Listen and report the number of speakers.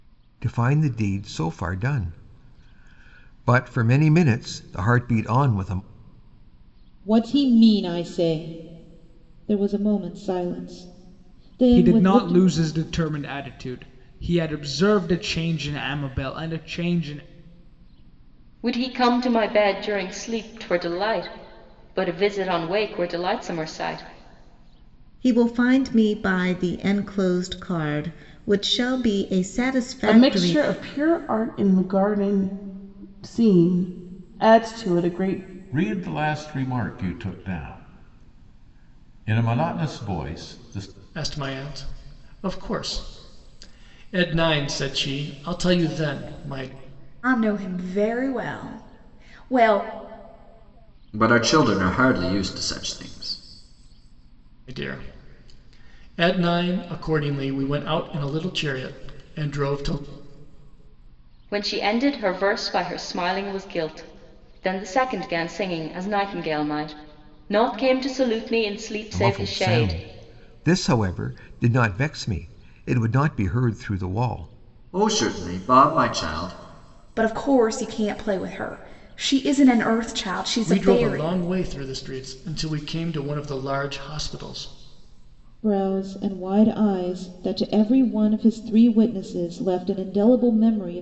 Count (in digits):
10